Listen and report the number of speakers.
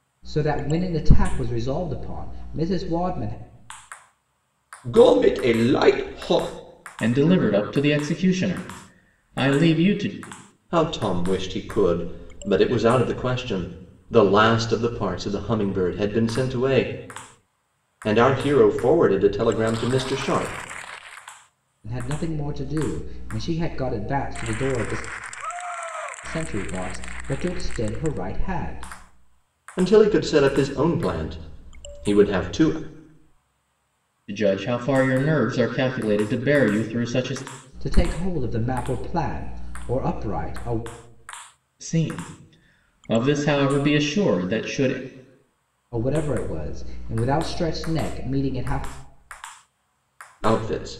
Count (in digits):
3